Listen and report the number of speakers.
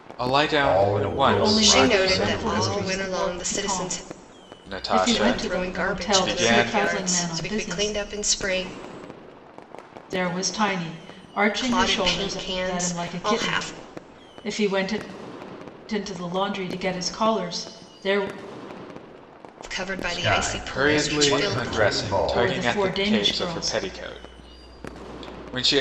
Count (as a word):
four